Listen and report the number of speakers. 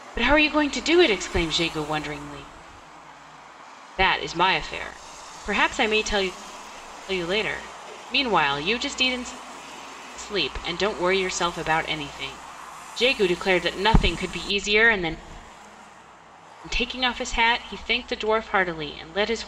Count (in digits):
1